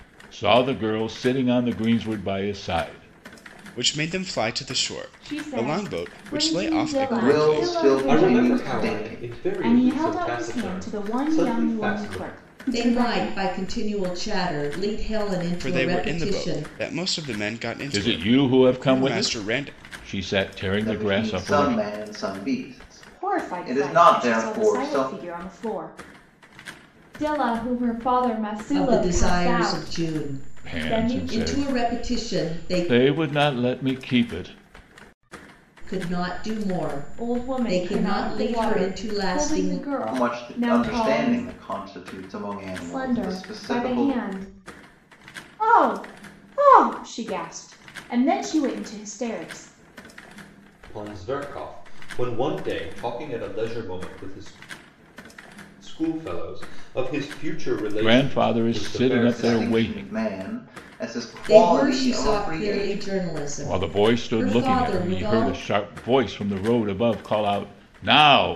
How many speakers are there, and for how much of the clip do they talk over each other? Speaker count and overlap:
7, about 43%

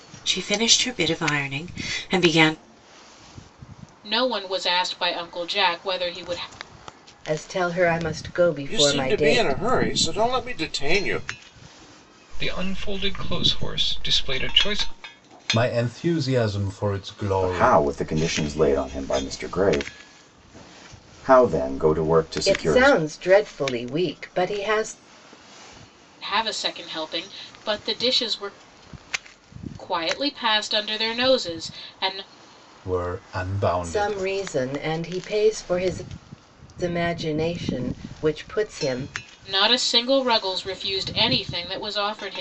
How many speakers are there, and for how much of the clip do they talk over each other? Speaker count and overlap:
7, about 6%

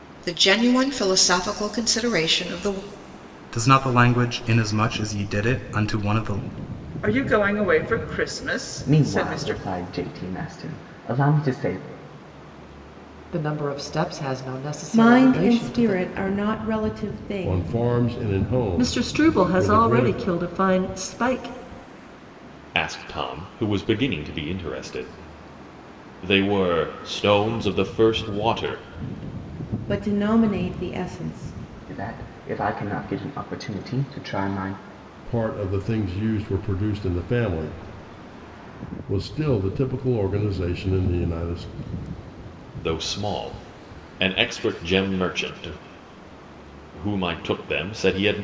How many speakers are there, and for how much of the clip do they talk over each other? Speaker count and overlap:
9, about 8%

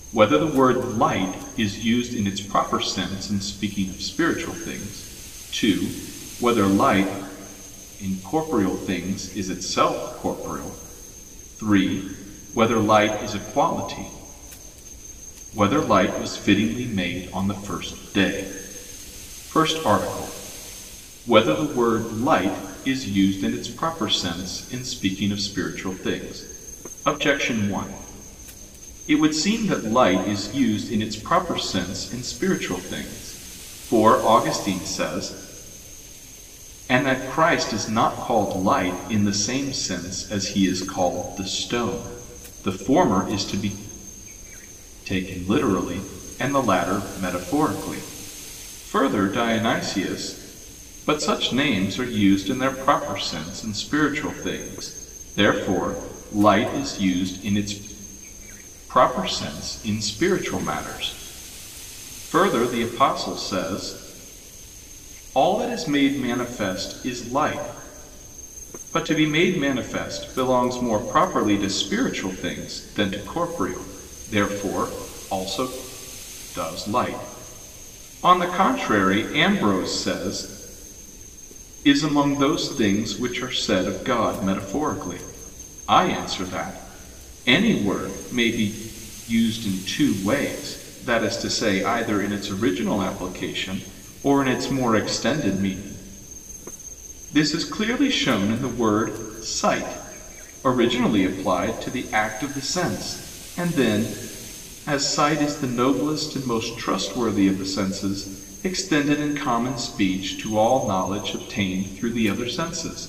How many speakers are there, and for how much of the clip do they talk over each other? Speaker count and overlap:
1, no overlap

